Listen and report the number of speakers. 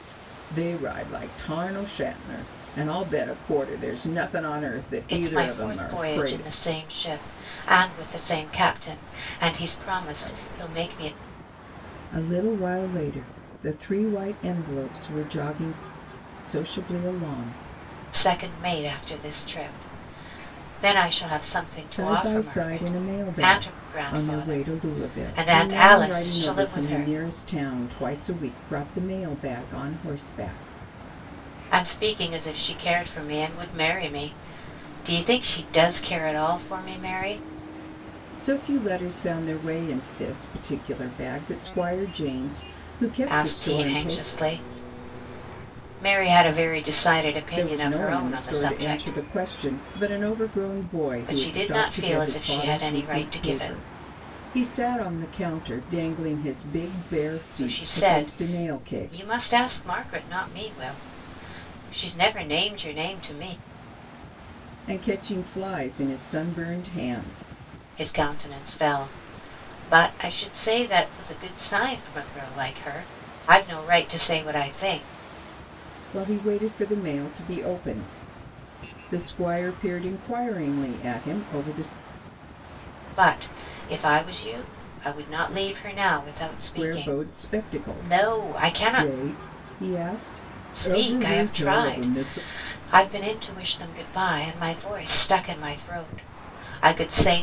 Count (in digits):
2